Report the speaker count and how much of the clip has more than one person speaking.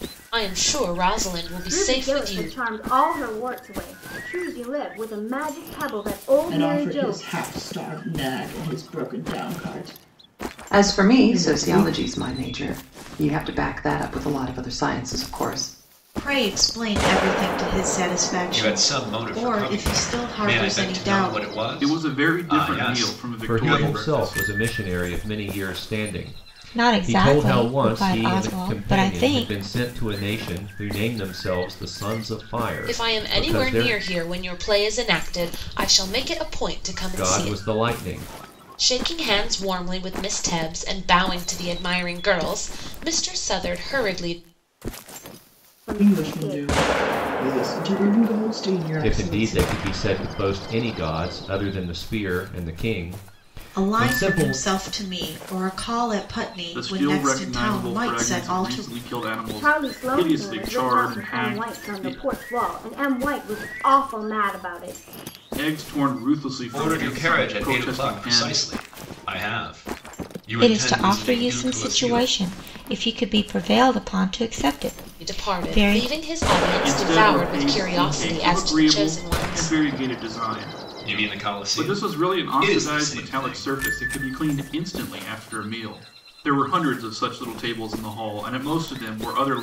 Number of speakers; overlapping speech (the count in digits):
9, about 33%